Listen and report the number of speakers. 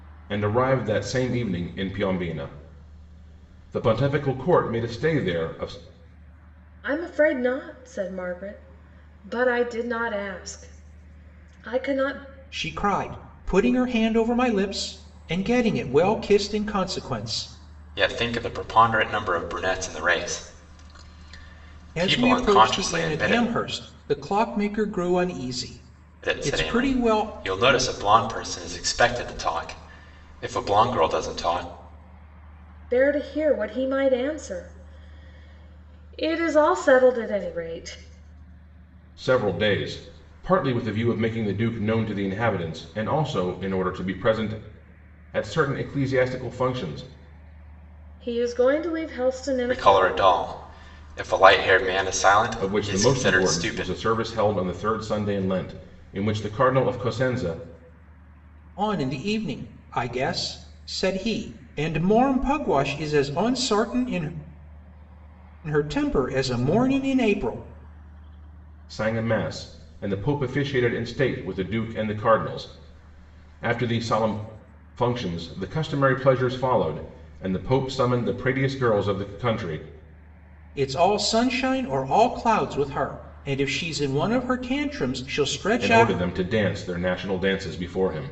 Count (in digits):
4